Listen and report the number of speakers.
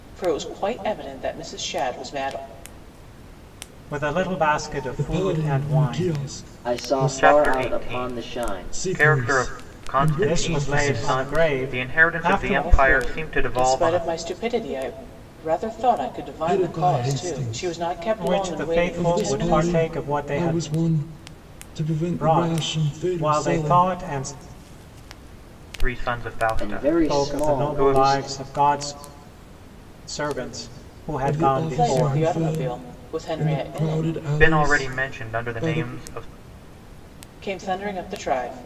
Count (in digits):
5